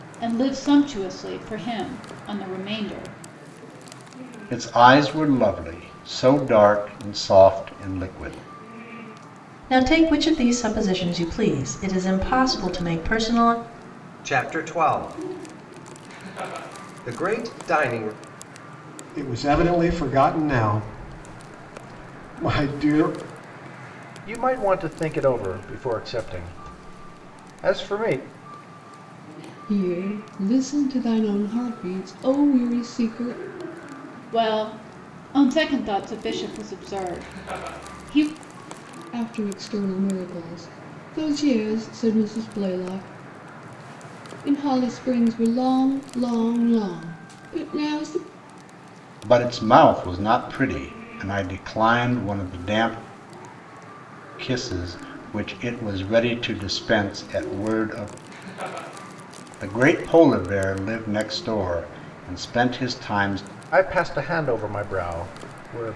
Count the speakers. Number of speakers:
7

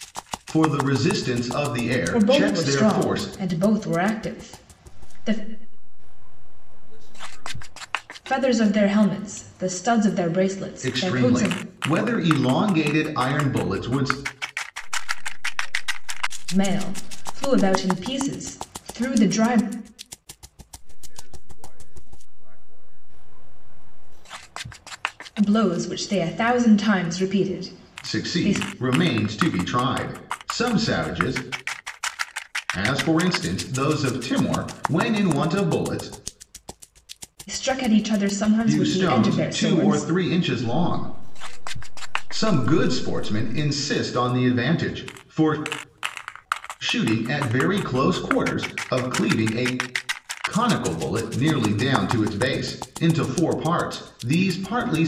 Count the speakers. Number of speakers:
3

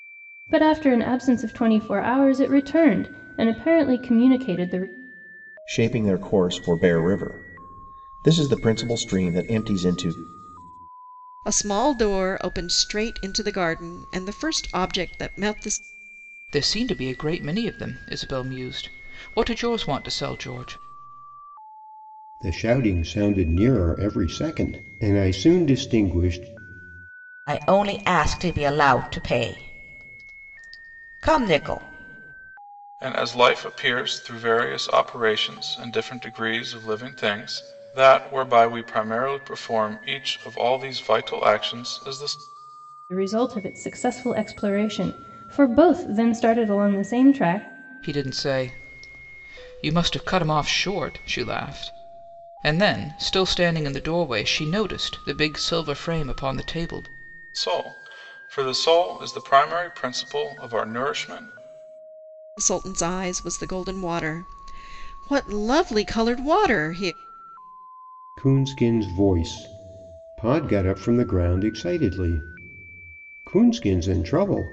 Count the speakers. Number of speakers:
7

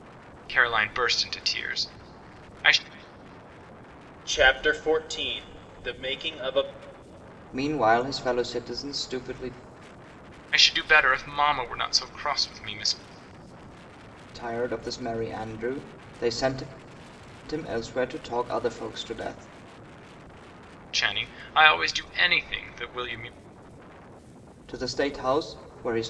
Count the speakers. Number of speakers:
3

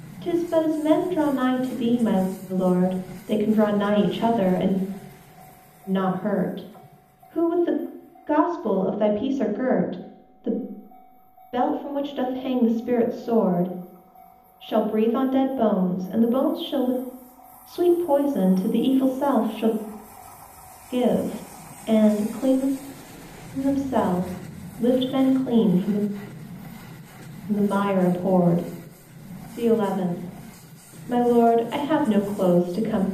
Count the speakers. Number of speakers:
1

